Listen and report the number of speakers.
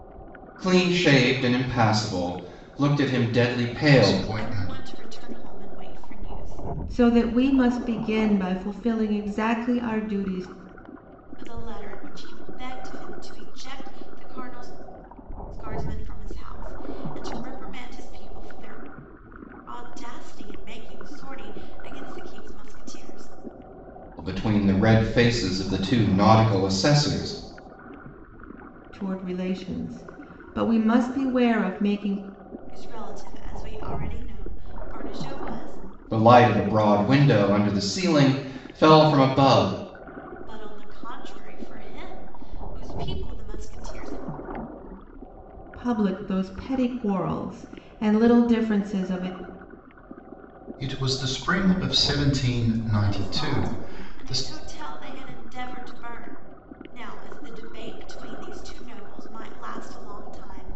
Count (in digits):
4